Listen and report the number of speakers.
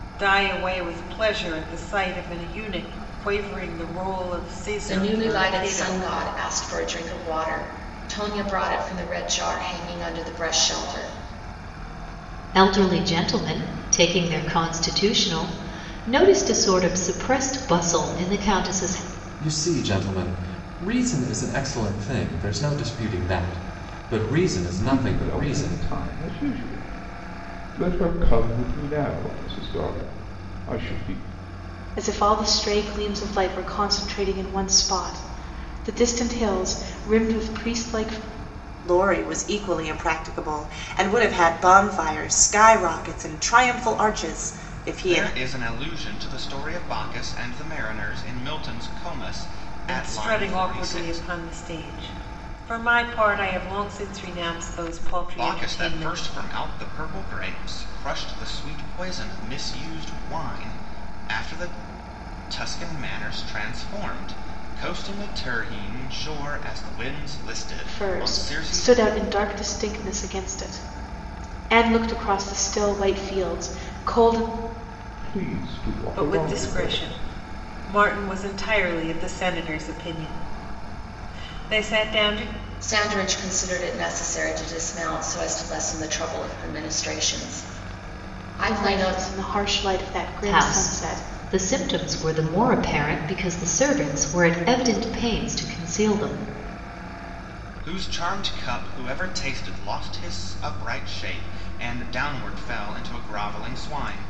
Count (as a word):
eight